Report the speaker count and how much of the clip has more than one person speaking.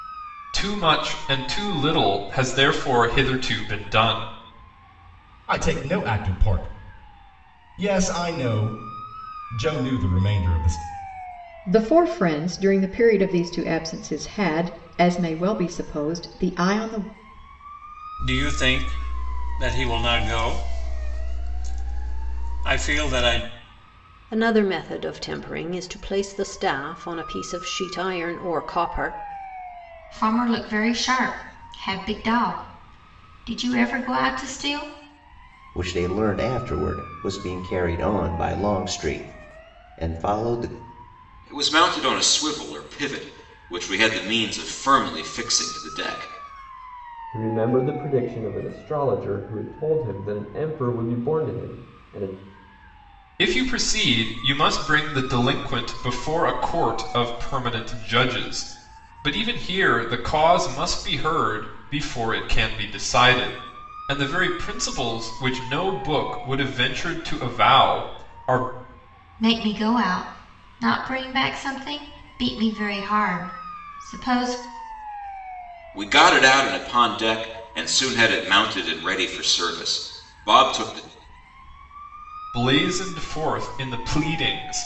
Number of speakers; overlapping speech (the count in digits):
9, no overlap